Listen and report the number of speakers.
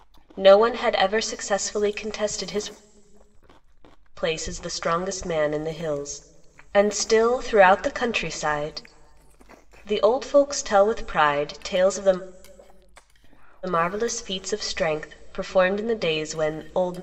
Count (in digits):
1